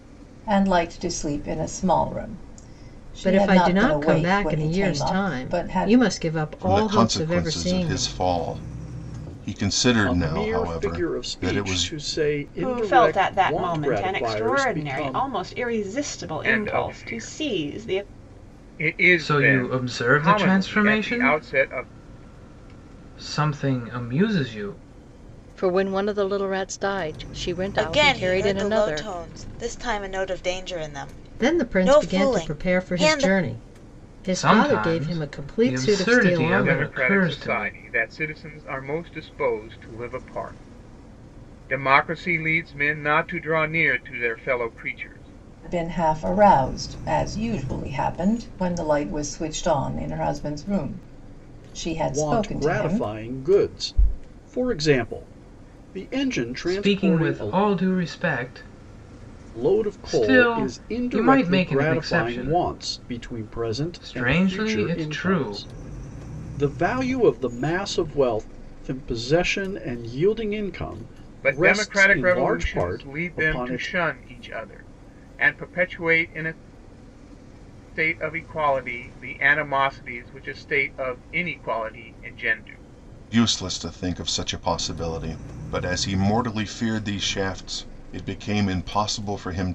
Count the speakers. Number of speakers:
nine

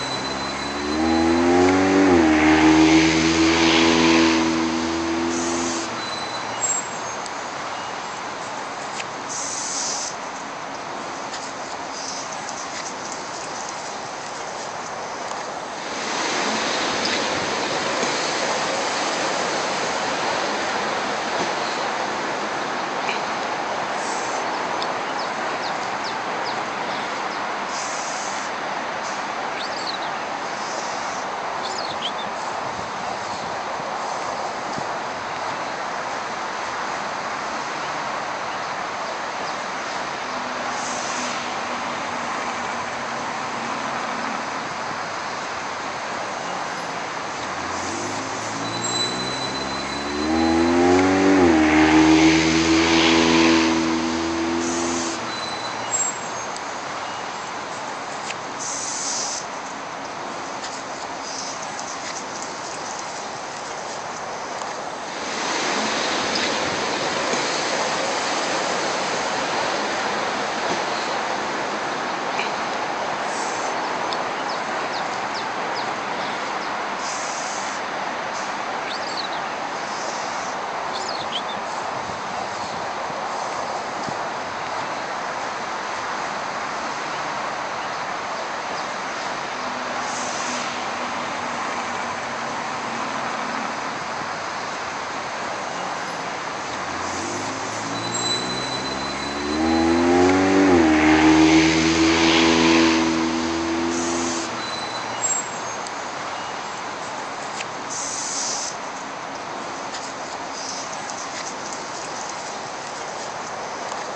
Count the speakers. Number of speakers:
zero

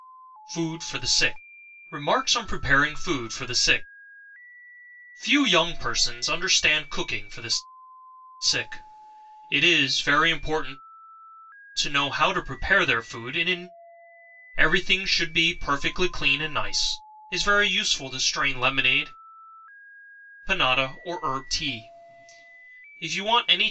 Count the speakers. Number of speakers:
one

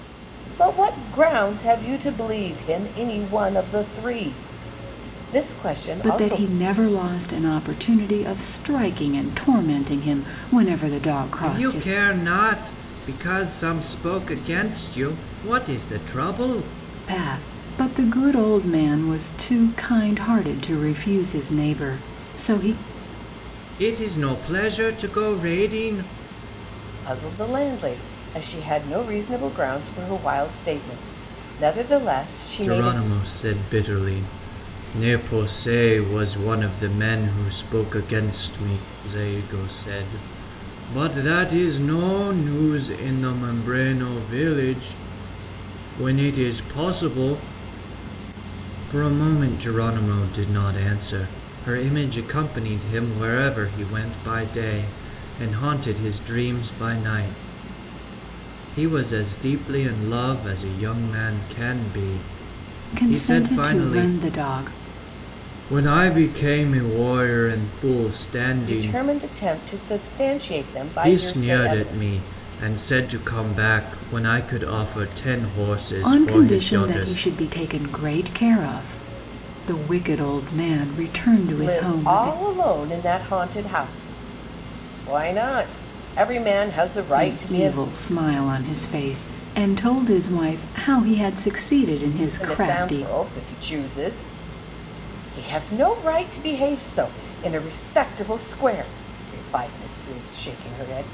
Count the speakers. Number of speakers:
three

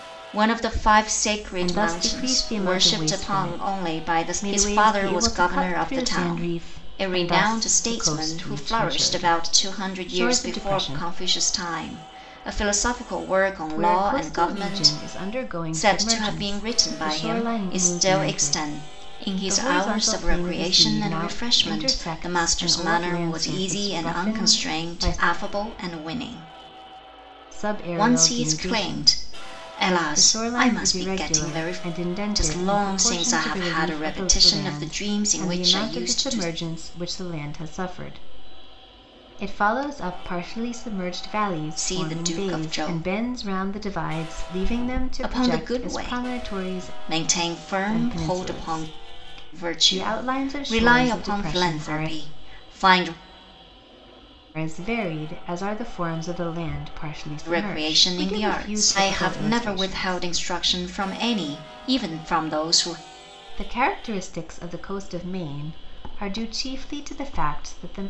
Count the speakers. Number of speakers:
two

